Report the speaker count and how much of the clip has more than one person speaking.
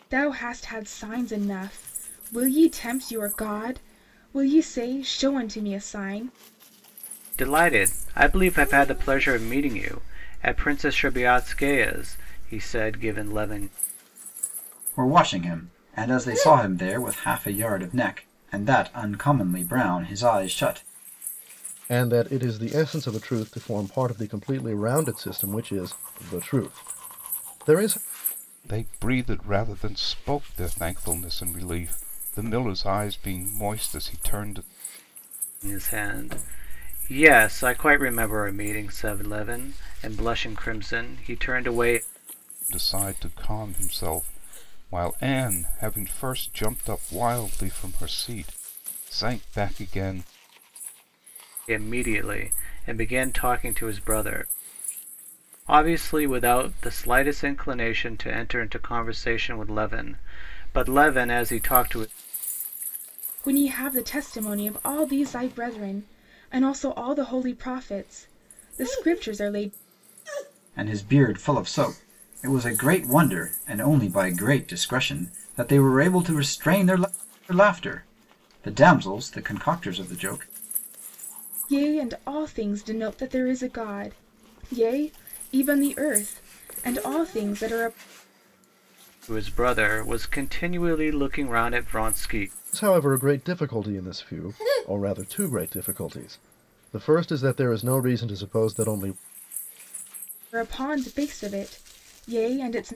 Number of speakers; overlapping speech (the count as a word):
five, no overlap